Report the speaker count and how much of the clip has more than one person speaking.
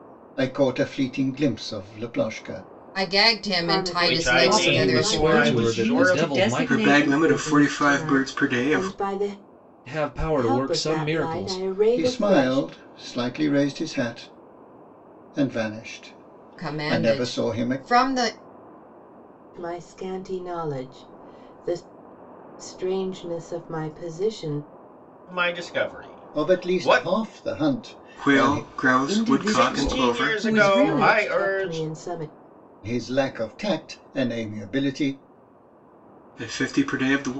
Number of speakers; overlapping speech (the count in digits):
7, about 35%